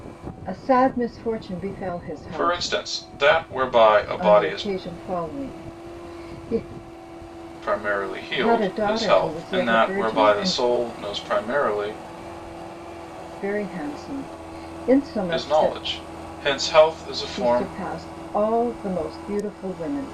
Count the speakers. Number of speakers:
2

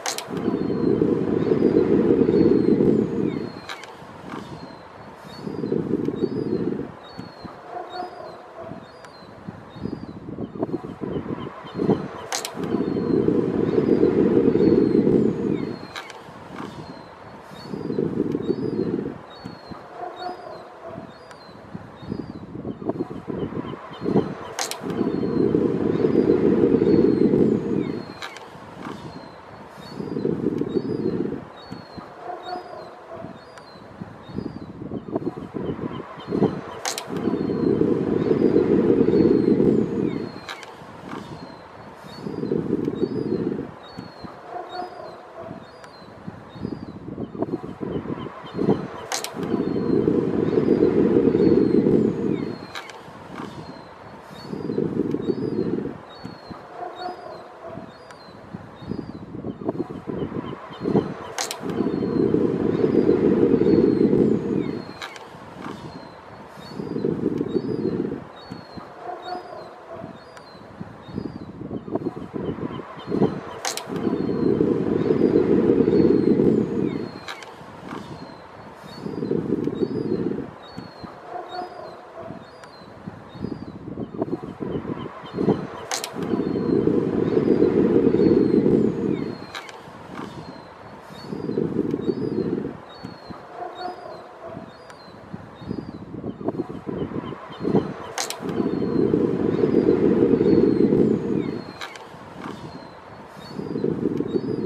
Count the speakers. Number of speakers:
0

